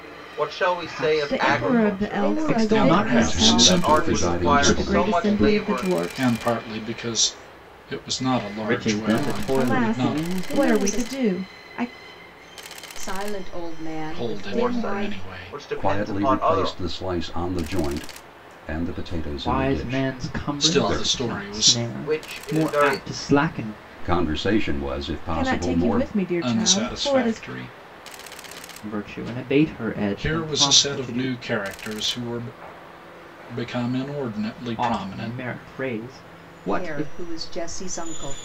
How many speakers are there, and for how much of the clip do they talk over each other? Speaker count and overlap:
6, about 48%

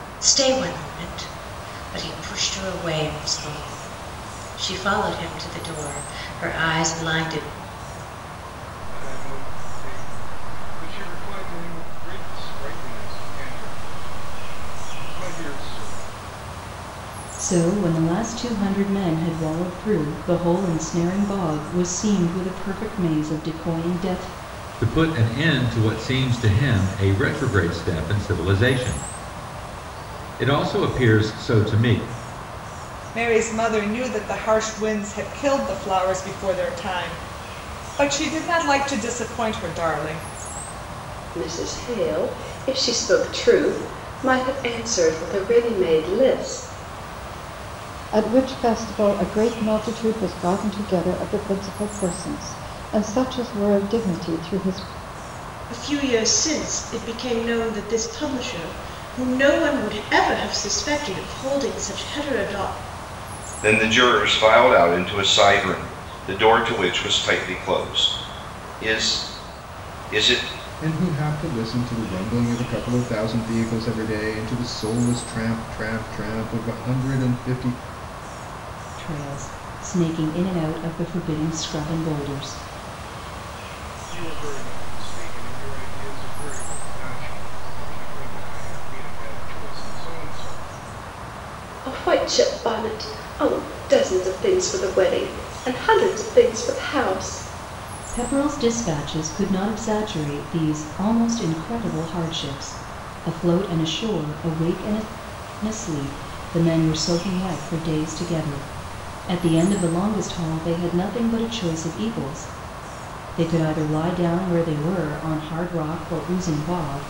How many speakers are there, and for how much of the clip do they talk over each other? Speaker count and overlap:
10, no overlap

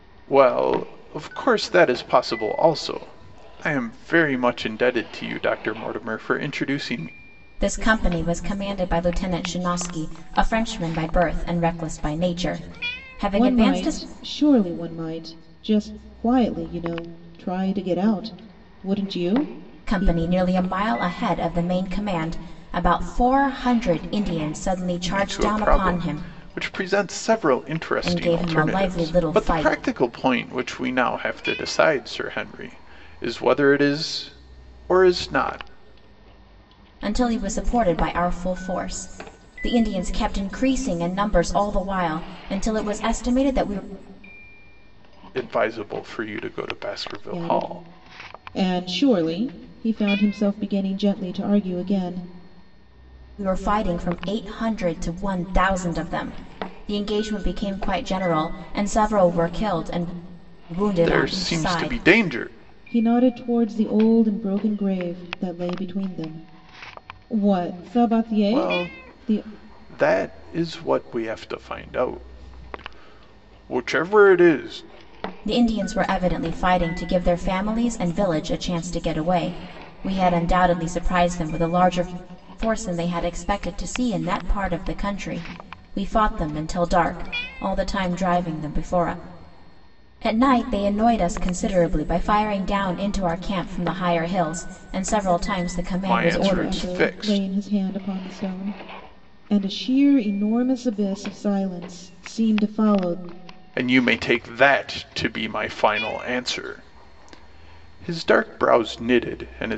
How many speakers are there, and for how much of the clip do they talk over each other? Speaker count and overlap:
3, about 7%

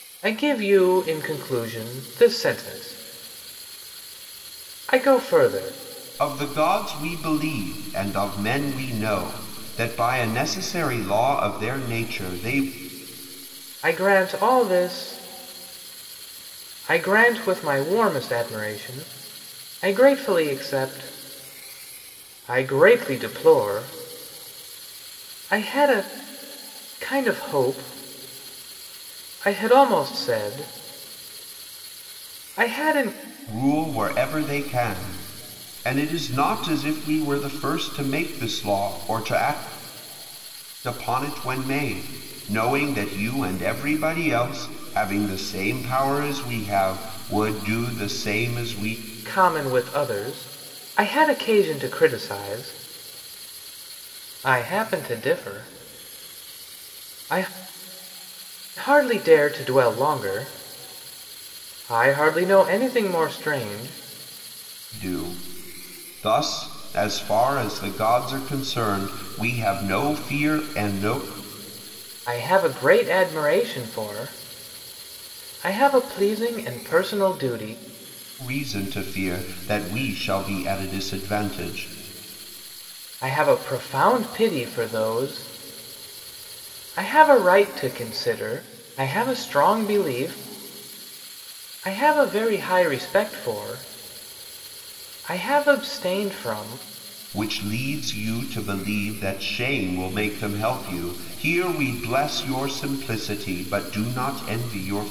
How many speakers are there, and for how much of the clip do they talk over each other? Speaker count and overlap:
2, no overlap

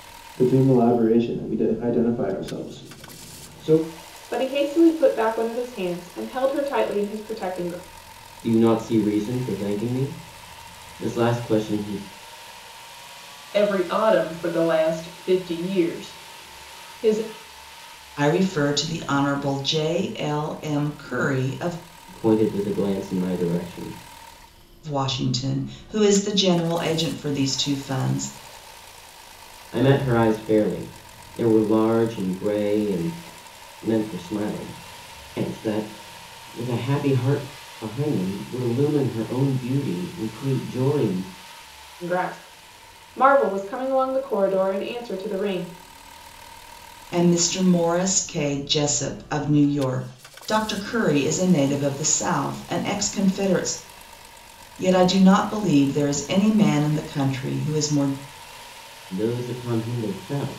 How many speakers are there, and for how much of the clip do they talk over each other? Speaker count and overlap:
5, no overlap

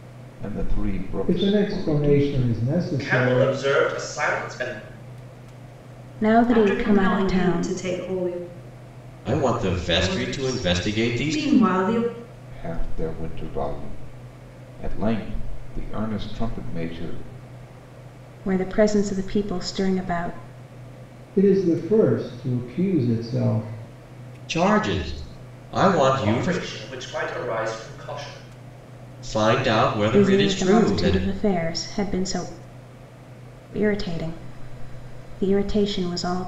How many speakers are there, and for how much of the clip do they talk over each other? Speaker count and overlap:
6, about 17%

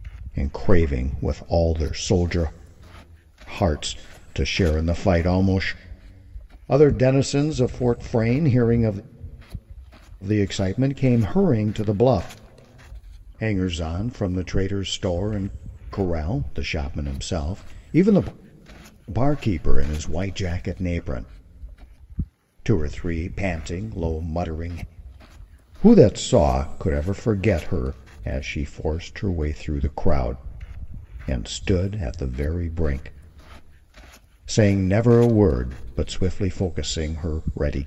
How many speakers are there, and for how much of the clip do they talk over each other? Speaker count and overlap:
1, no overlap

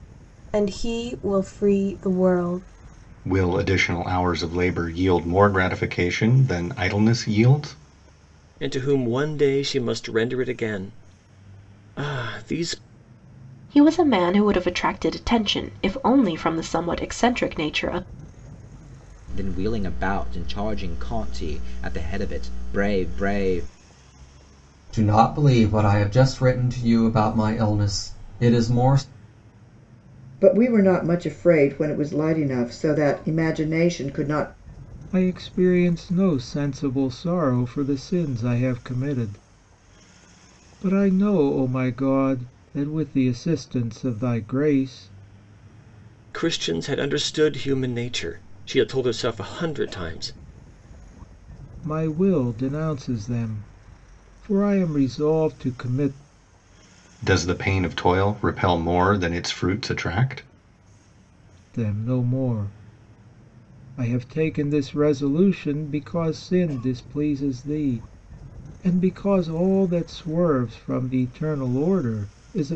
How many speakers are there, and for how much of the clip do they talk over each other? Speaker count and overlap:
8, no overlap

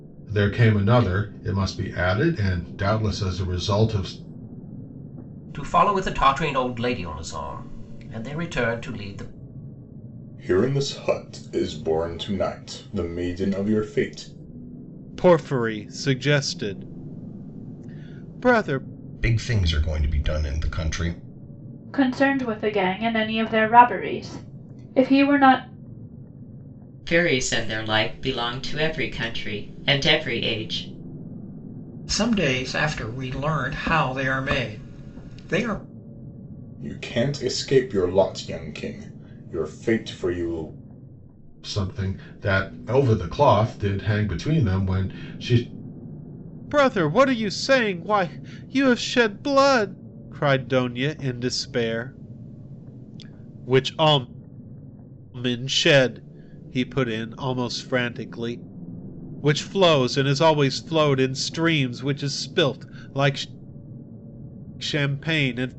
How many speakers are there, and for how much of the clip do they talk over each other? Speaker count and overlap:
8, no overlap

